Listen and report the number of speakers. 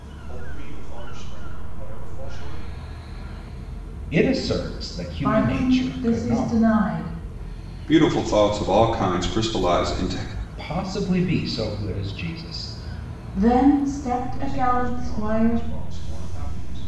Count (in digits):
4